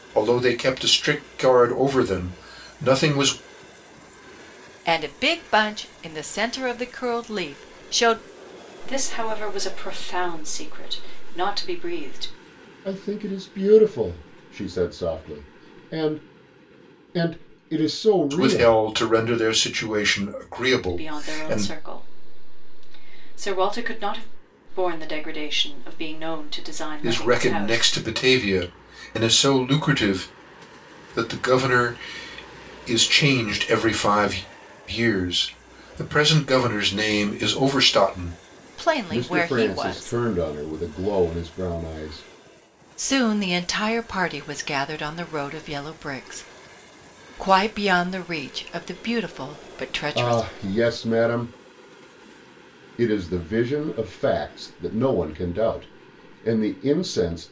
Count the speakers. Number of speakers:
four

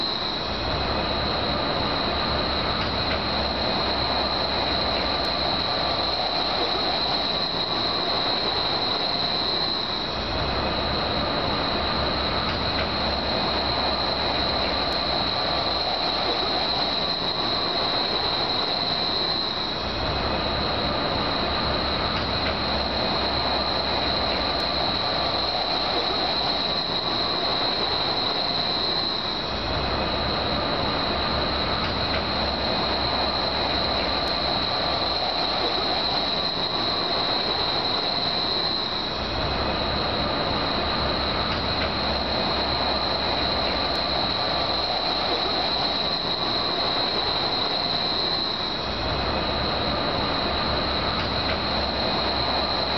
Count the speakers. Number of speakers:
zero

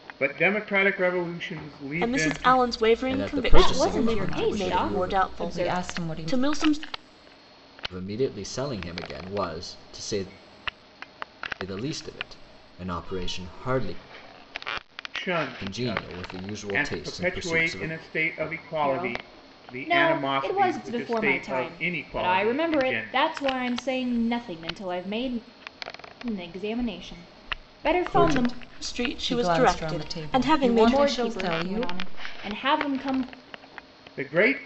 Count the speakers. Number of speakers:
five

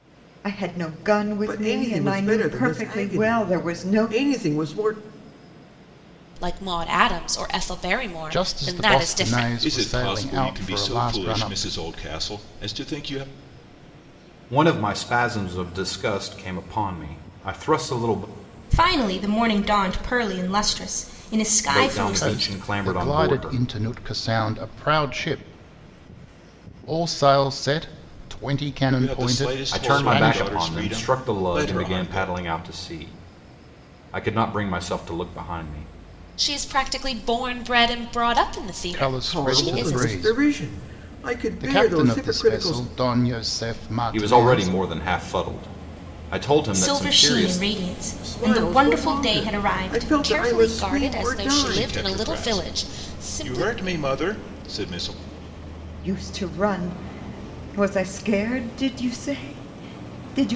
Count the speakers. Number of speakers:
seven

